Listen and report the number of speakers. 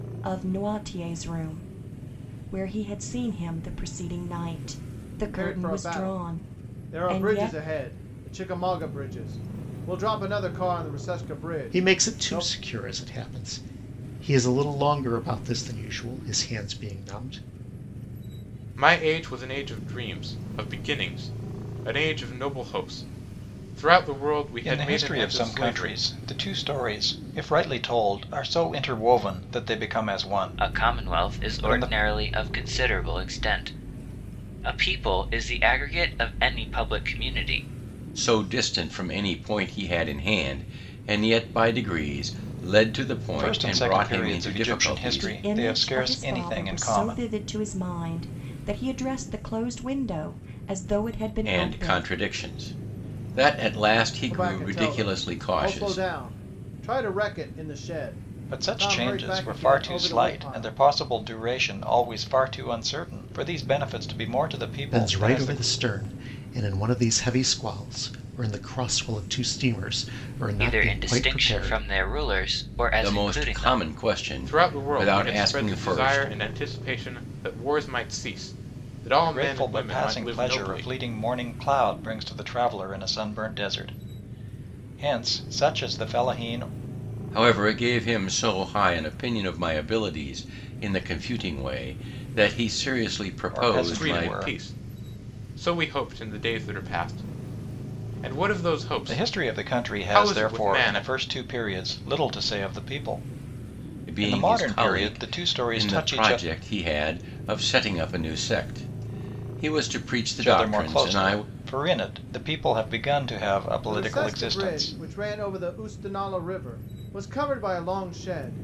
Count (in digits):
7